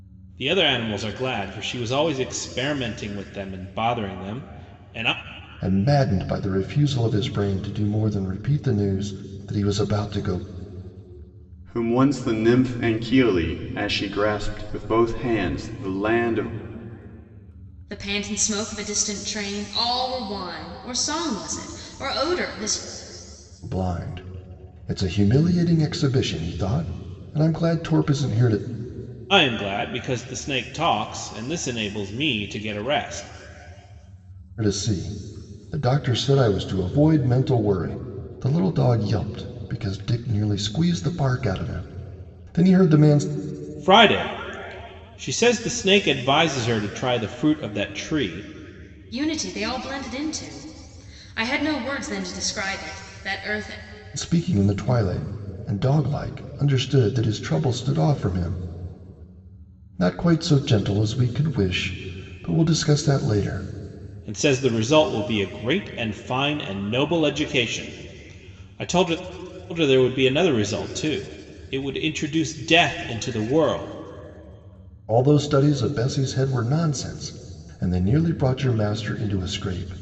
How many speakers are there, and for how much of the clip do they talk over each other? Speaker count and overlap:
4, no overlap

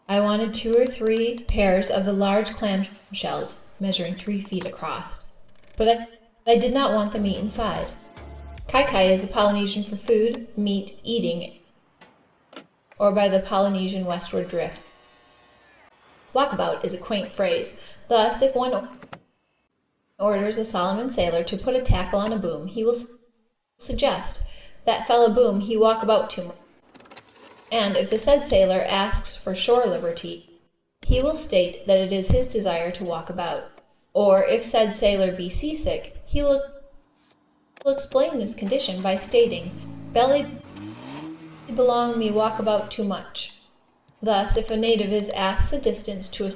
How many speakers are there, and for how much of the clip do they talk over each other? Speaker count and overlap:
1, no overlap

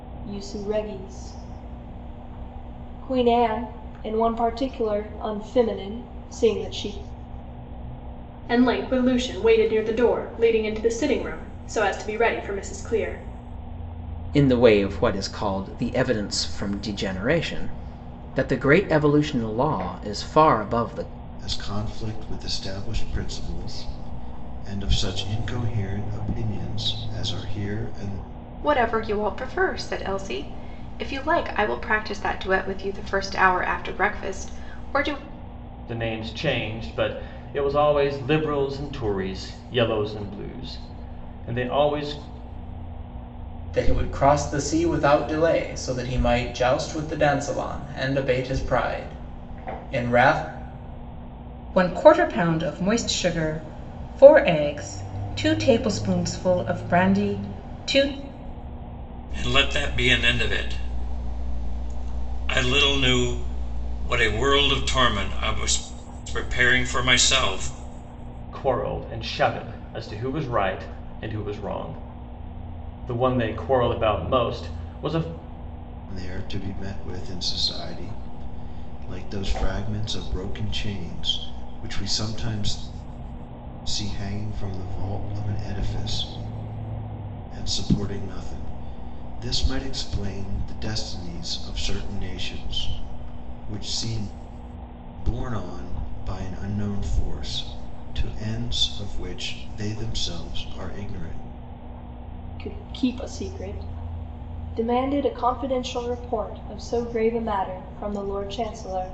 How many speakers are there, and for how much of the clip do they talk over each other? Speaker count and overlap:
9, no overlap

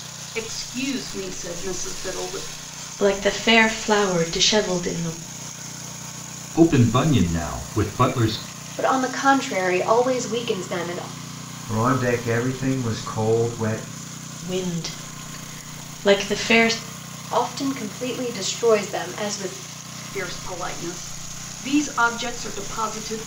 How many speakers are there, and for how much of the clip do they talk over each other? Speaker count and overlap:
5, no overlap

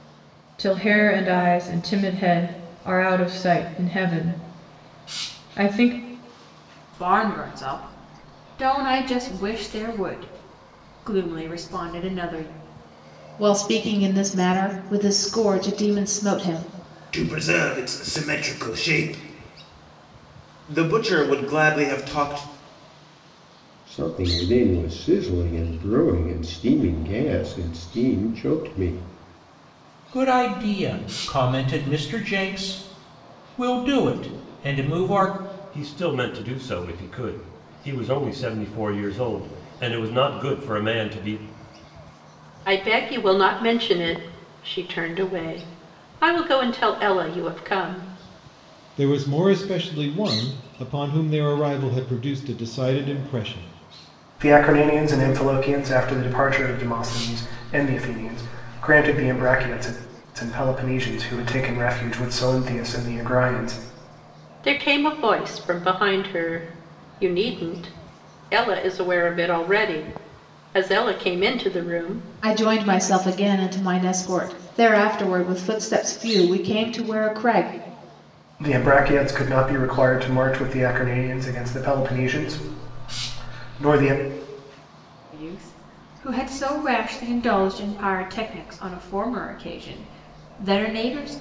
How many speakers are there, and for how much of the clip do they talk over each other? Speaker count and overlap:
10, no overlap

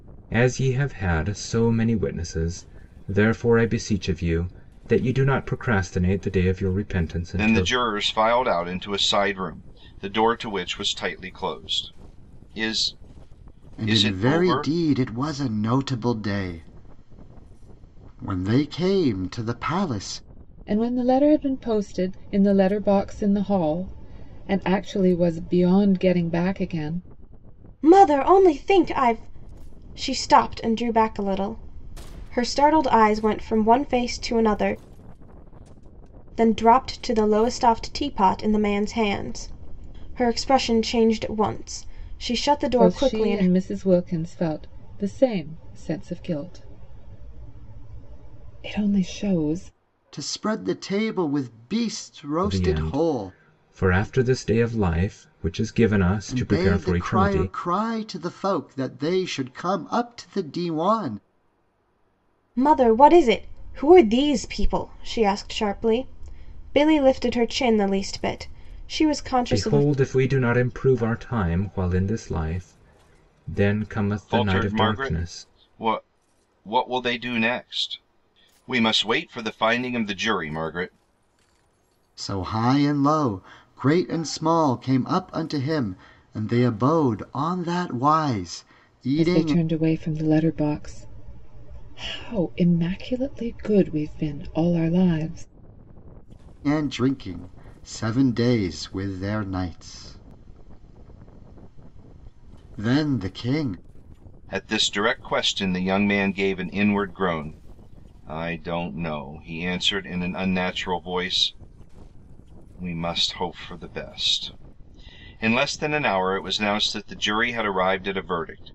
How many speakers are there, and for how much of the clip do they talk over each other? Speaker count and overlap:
5, about 5%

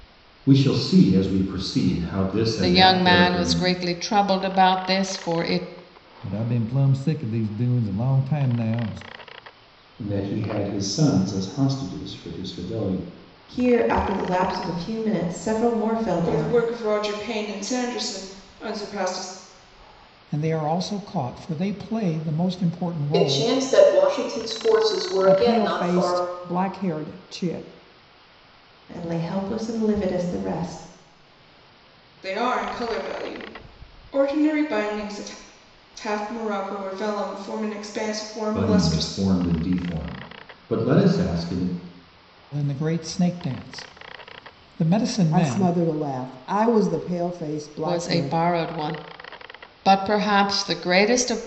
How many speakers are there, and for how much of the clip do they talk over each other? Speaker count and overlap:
9, about 9%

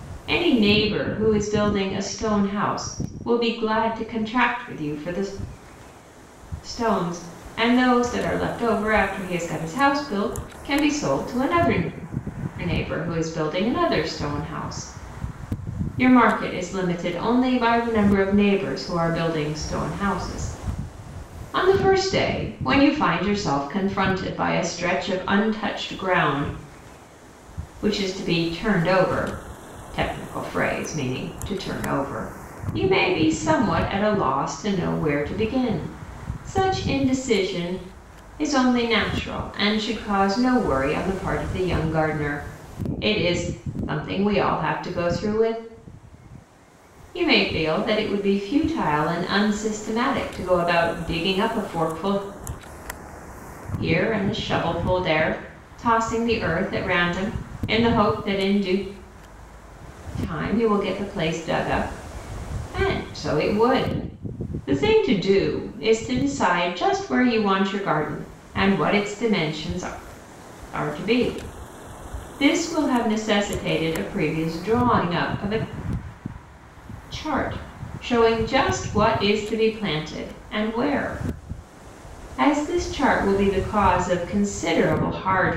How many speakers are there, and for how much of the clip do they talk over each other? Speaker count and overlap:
1, no overlap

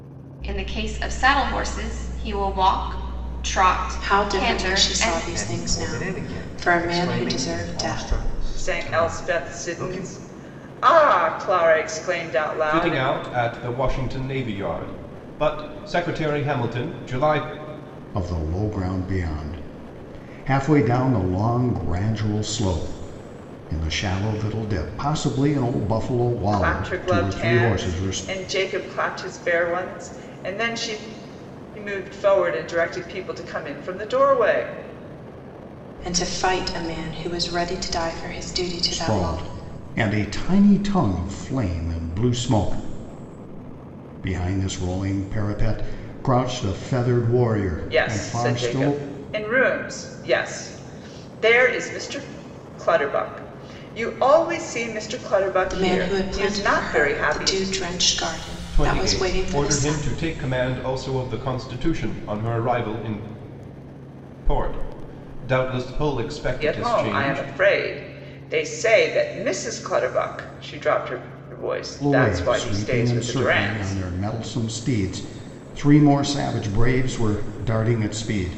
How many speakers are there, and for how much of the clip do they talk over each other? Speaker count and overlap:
6, about 20%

